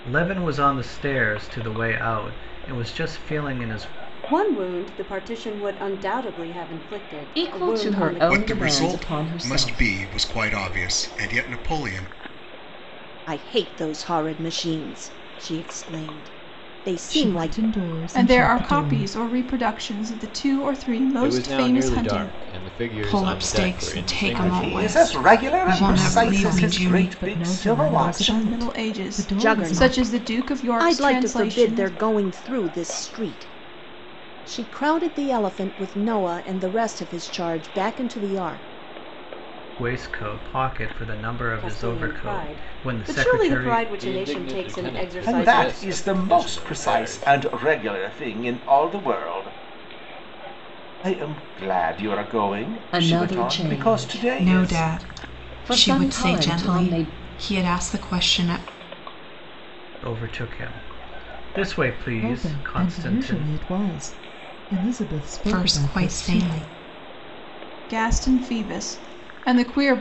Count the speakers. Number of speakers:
ten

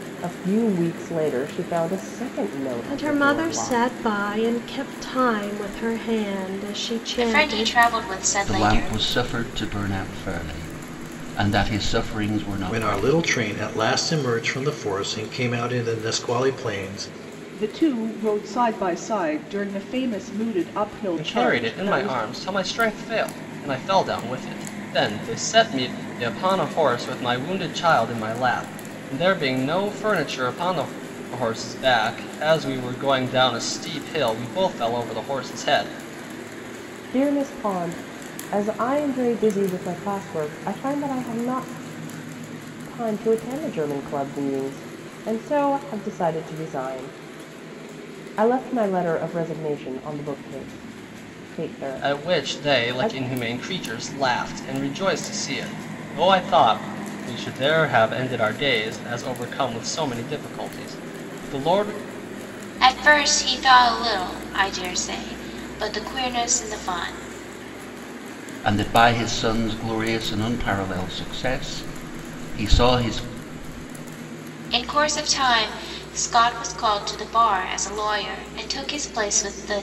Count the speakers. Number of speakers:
seven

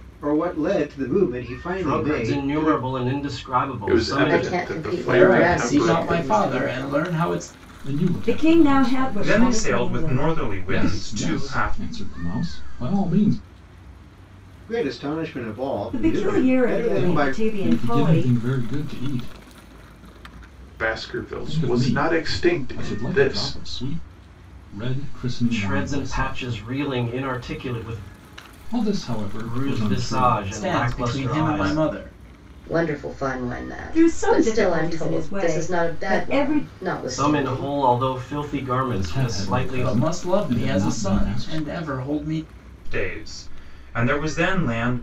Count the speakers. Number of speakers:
eight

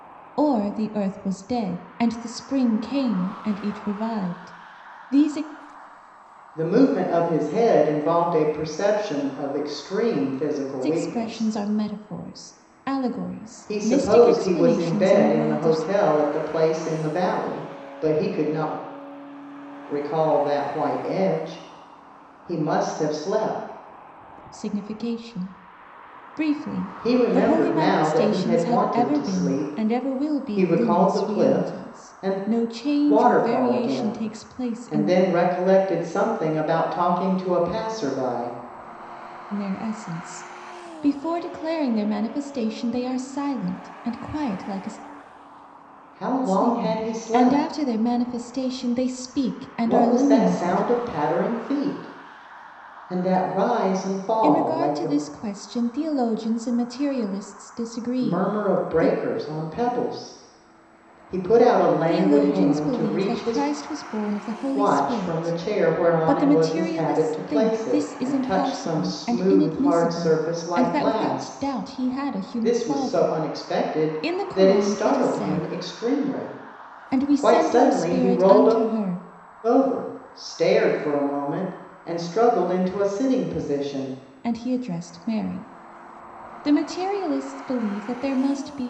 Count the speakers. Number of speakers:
two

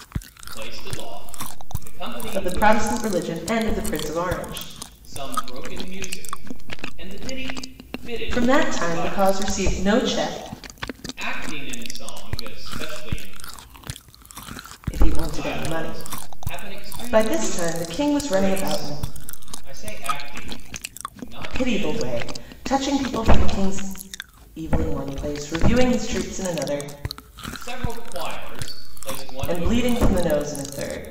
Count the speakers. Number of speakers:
two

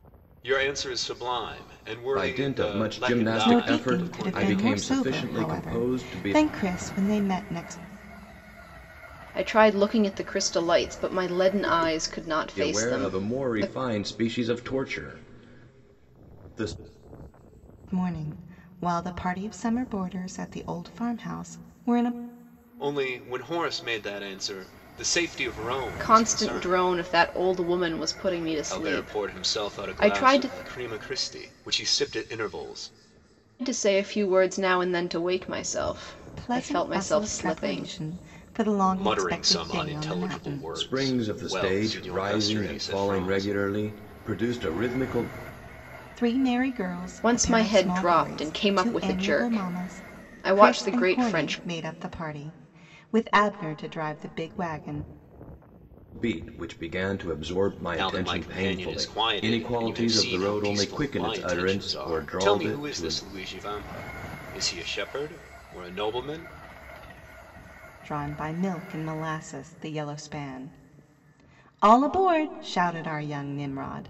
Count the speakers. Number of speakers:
four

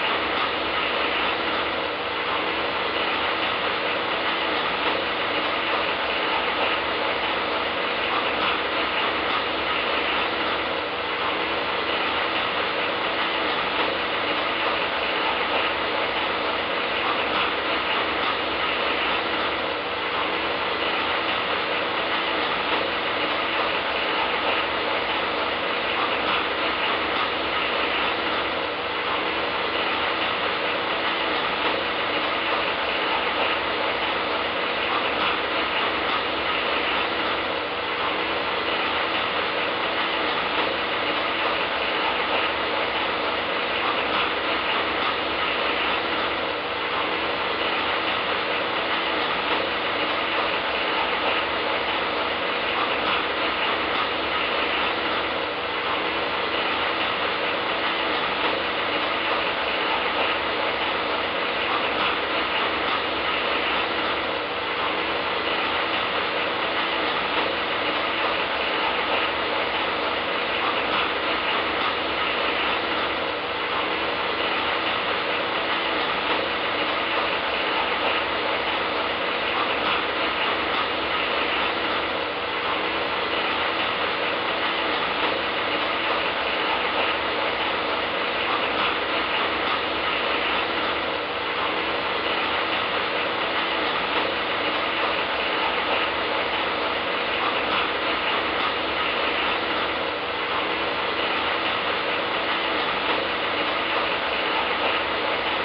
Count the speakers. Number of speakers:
zero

